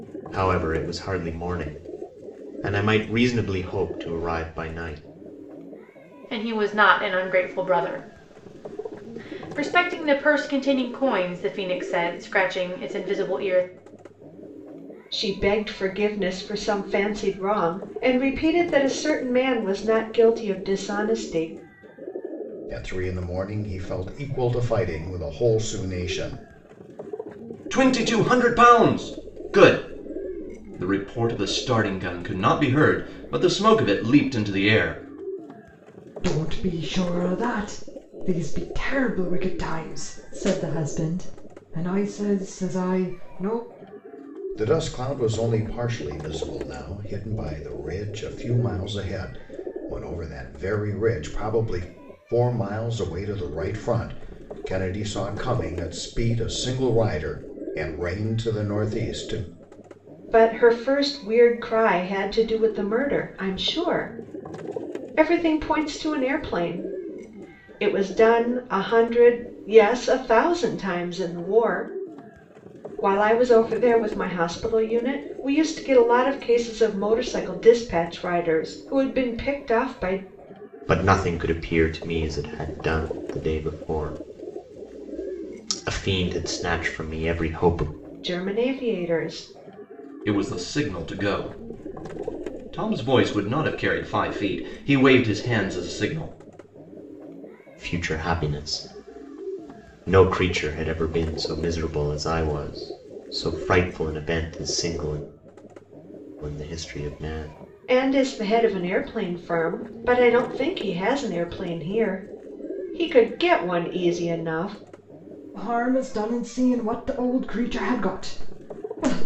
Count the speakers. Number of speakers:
6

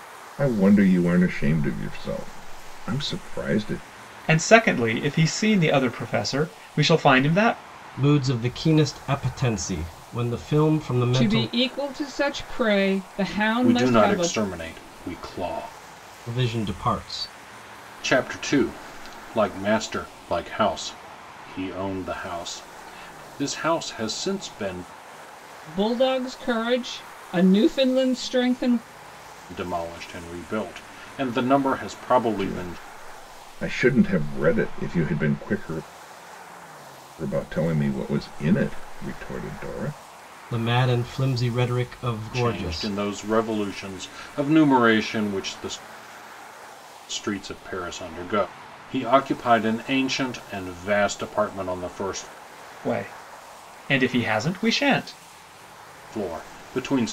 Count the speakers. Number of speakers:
5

